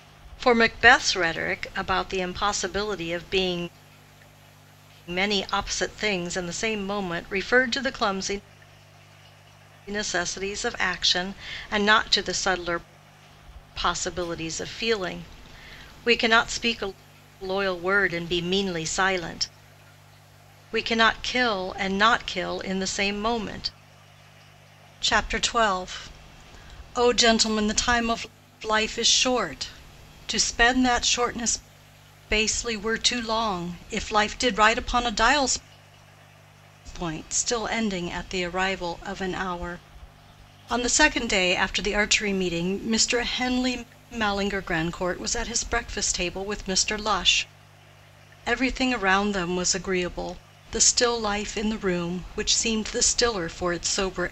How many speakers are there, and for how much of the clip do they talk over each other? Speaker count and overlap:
1, no overlap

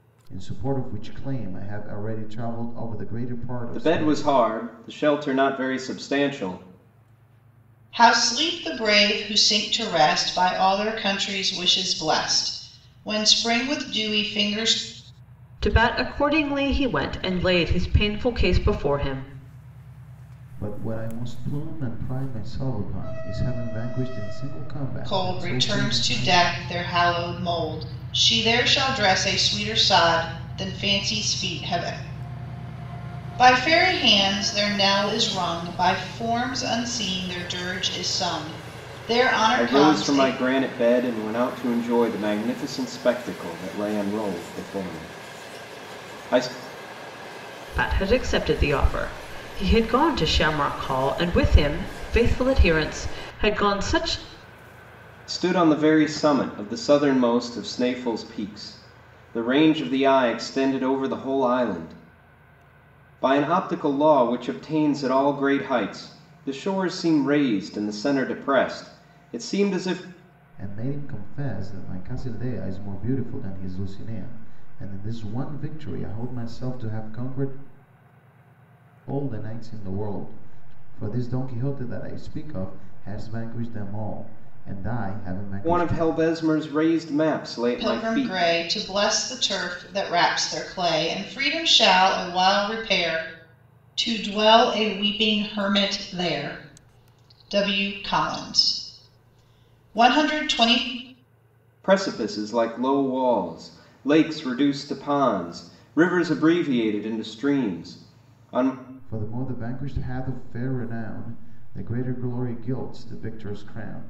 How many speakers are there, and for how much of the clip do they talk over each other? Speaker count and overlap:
4, about 4%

